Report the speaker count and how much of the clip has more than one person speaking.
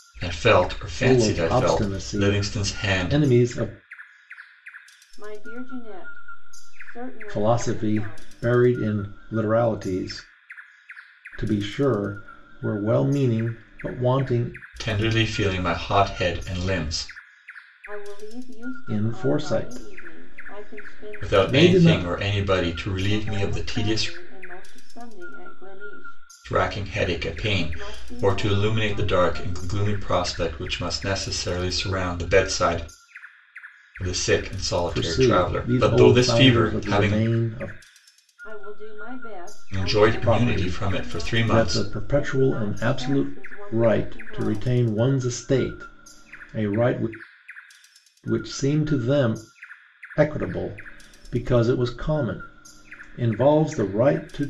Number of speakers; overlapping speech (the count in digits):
3, about 32%